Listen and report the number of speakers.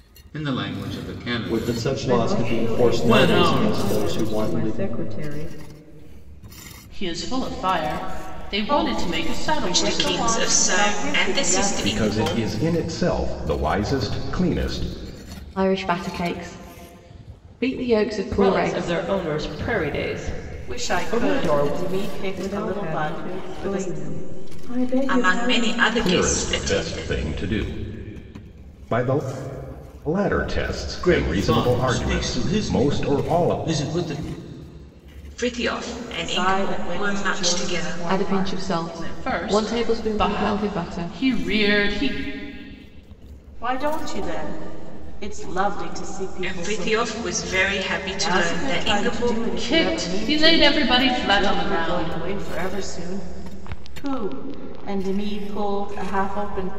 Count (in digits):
9